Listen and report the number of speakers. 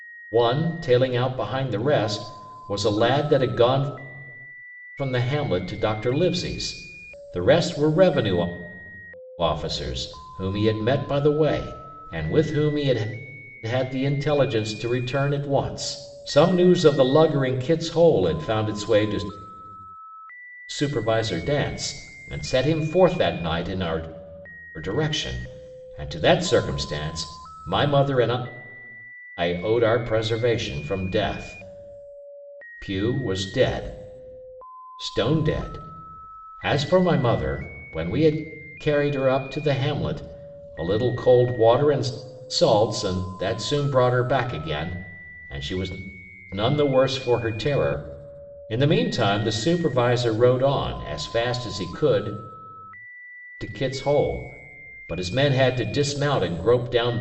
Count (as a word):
one